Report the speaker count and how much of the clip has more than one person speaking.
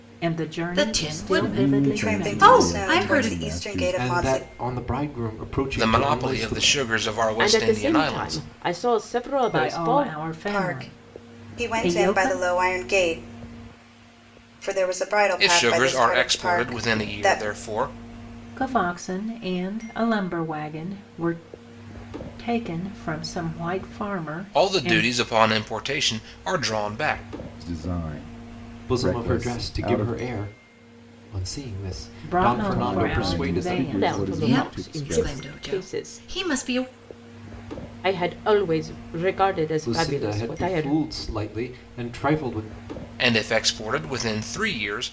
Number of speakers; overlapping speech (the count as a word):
seven, about 39%